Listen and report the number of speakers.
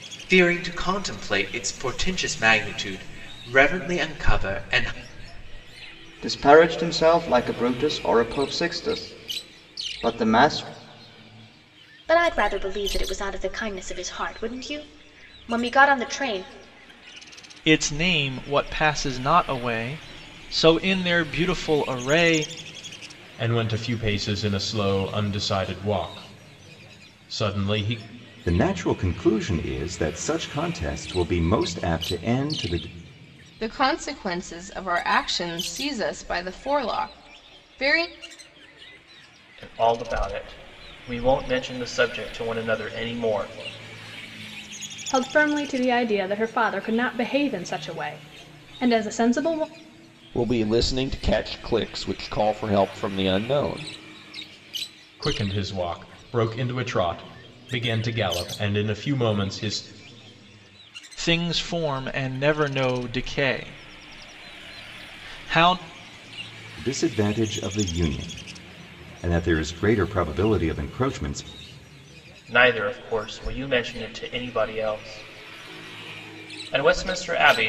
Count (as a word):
ten